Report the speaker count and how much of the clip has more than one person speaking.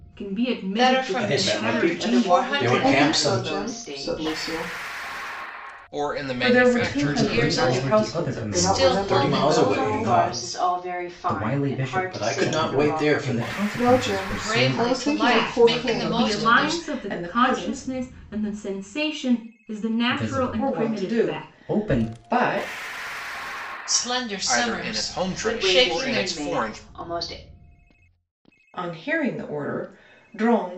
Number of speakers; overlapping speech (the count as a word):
eight, about 63%